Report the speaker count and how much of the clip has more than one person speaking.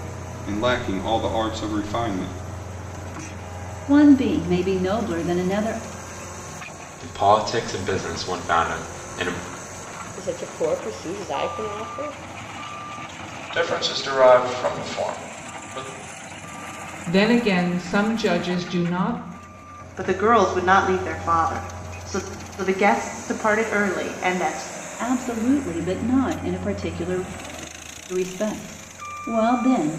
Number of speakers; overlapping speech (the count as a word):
seven, no overlap